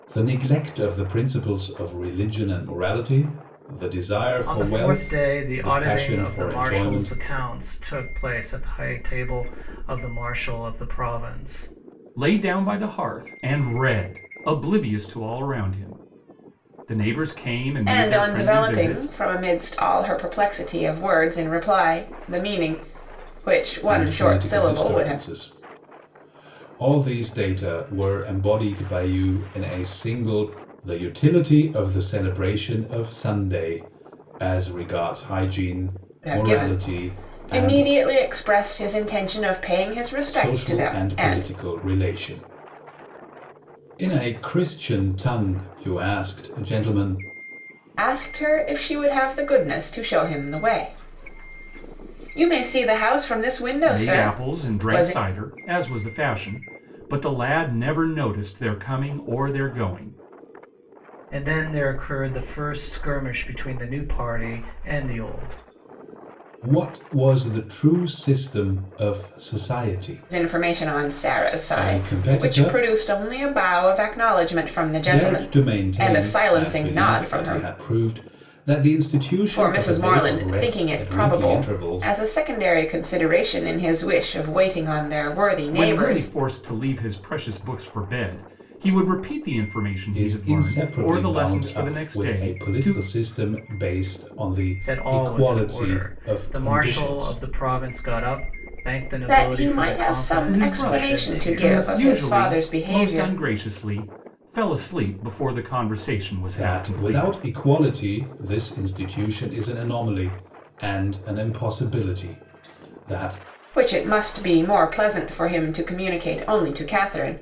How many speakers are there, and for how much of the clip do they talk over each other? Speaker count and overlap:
four, about 24%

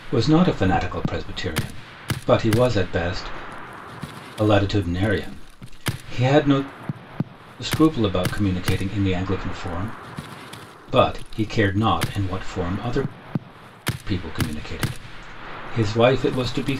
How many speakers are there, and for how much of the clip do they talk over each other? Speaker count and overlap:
one, no overlap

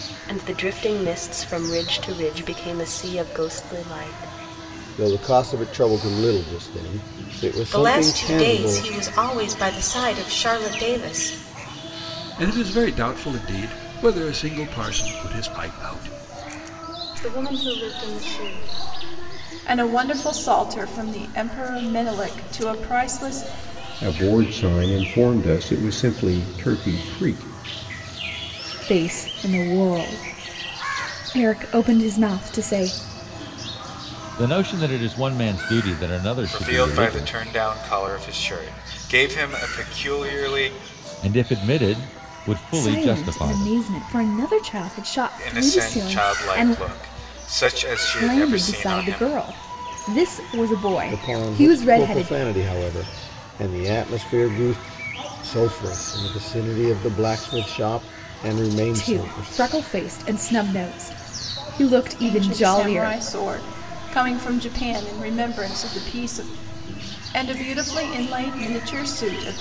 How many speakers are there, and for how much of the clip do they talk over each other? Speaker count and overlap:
ten, about 12%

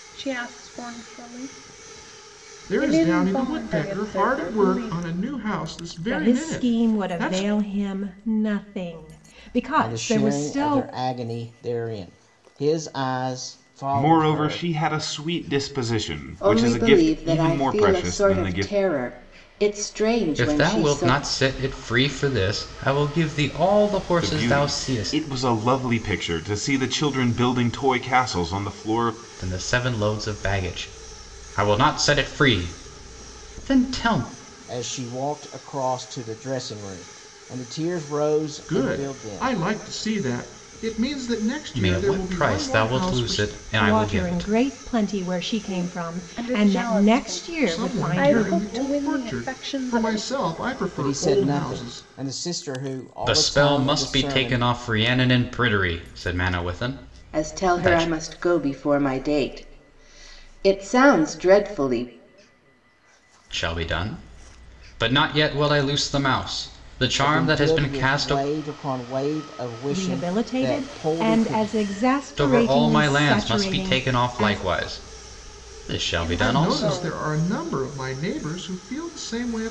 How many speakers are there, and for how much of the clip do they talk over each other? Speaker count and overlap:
seven, about 35%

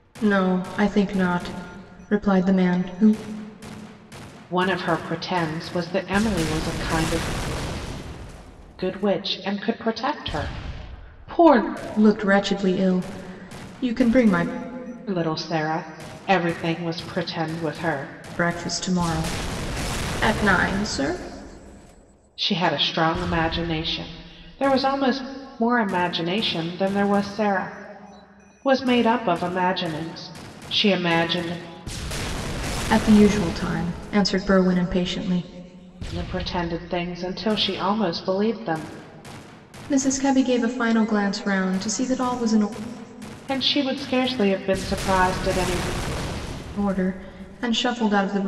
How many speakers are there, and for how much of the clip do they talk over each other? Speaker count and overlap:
two, no overlap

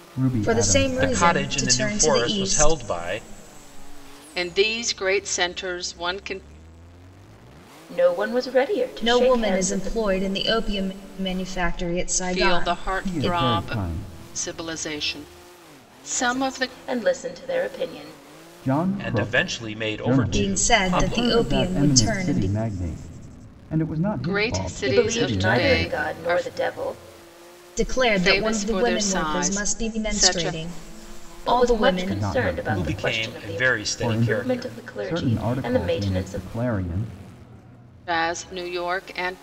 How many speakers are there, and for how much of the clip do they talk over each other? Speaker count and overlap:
five, about 48%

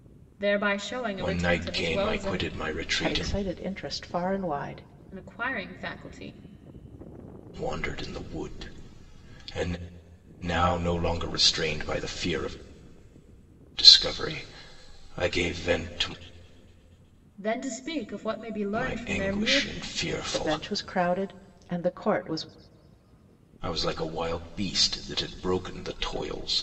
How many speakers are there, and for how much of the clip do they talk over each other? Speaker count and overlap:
three, about 12%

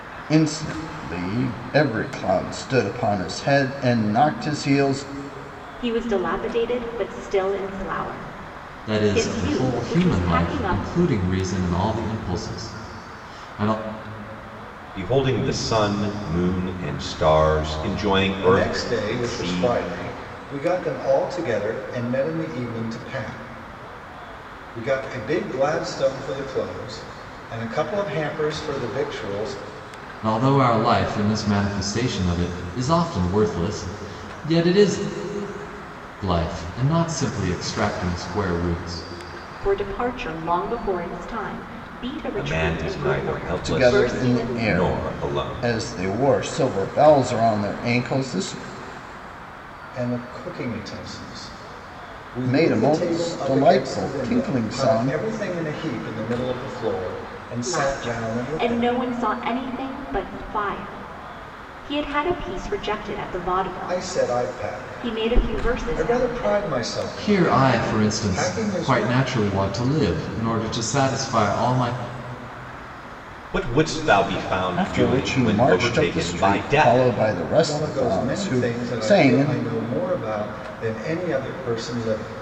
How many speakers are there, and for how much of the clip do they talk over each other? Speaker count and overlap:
five, about 24%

